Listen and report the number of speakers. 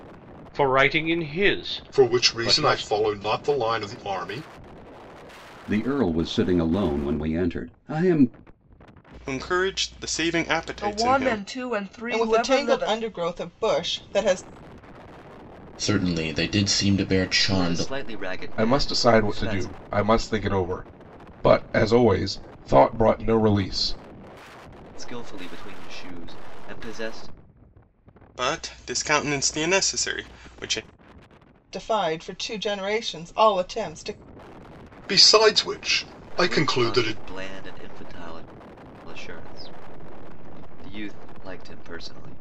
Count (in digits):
9